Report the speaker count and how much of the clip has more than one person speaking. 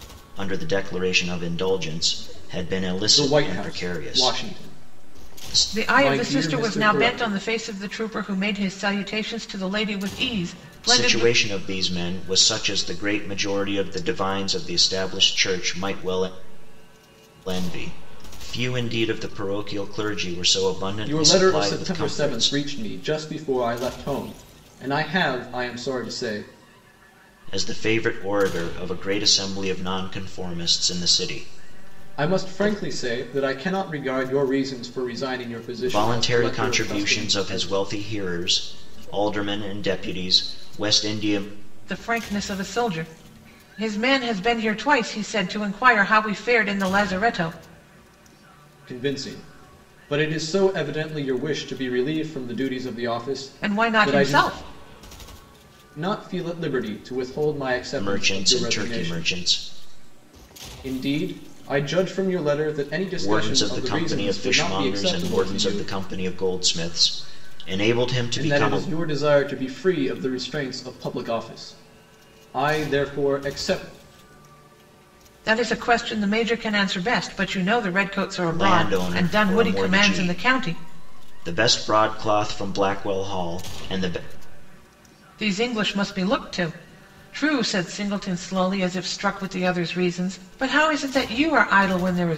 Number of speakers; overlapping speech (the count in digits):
3, about 18%